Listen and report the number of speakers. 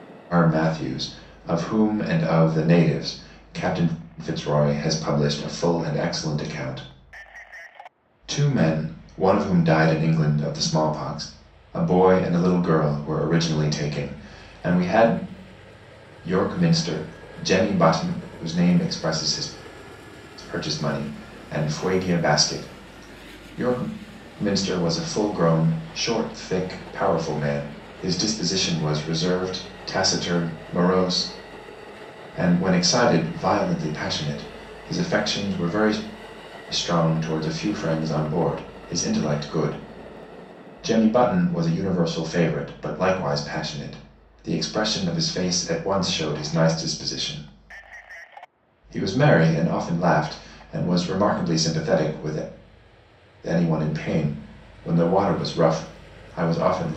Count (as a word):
one